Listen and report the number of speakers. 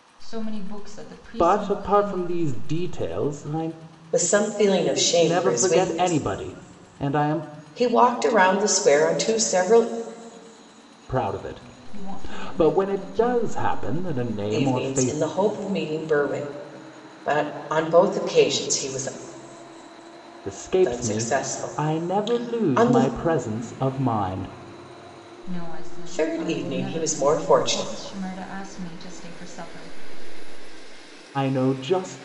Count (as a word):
three